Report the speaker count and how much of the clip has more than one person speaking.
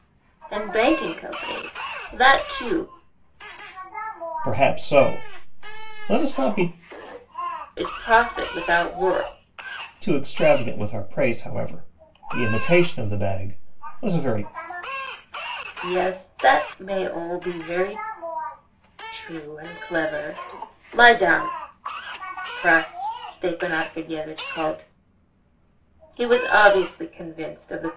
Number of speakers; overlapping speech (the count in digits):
2, no overlap